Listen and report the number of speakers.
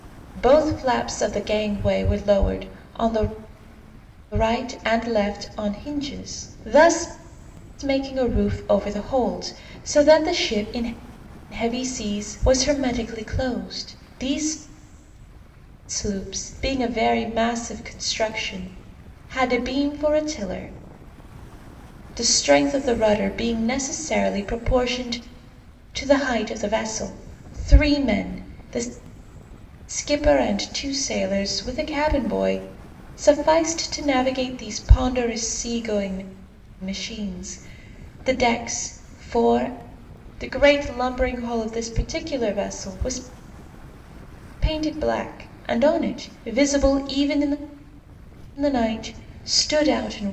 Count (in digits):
1